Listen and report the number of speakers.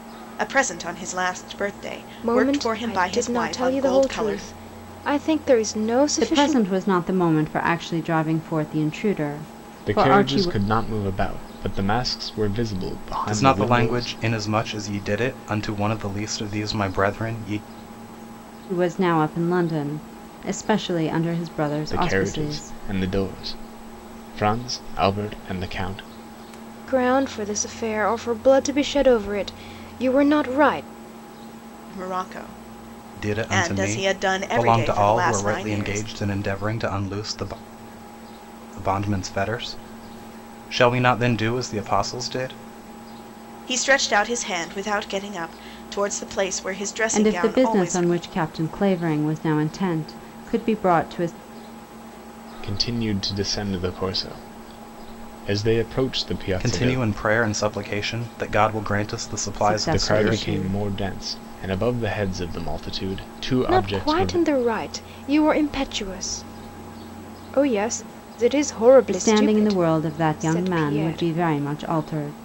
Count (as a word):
five